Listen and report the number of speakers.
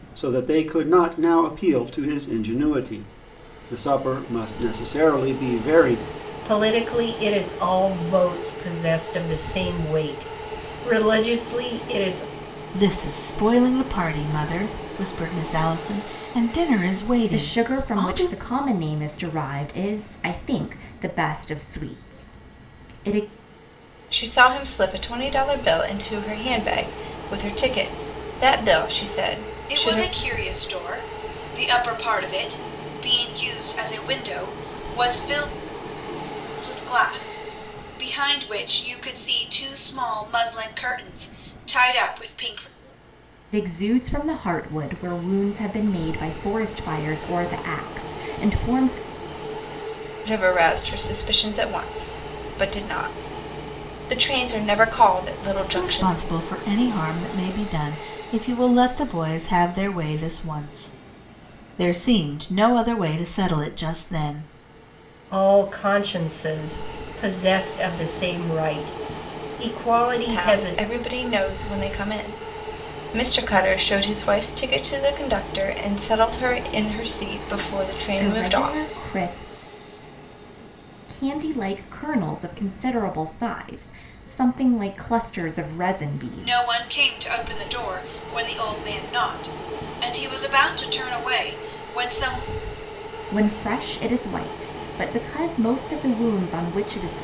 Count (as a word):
six